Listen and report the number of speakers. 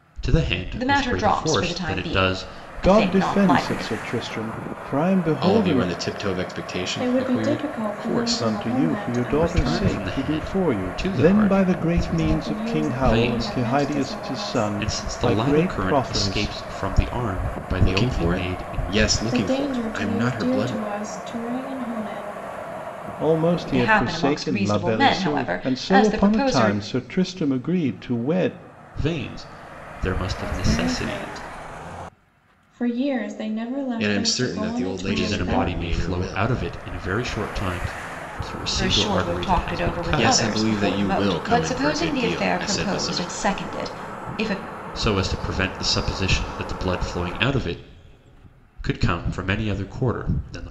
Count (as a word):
five